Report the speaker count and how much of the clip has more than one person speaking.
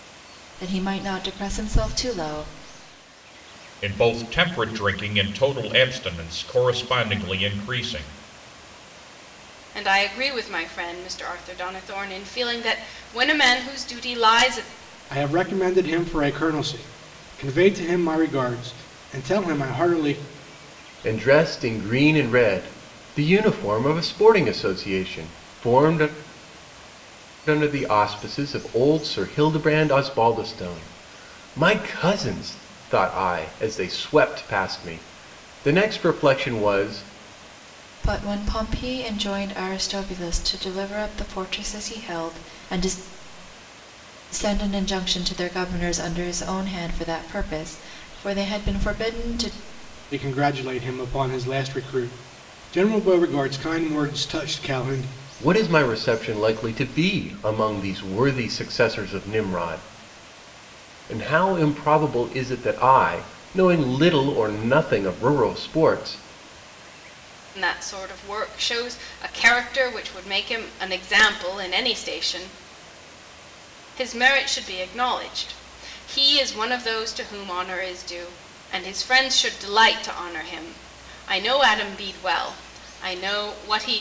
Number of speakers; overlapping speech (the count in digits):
5, no overlap